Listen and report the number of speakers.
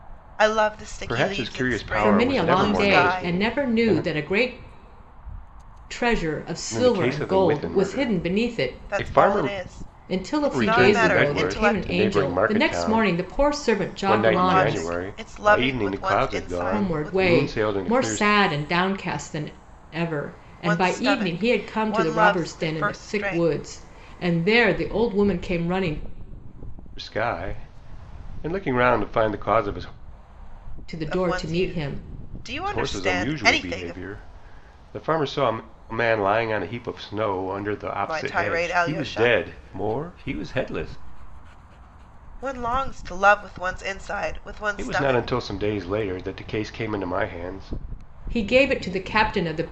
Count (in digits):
3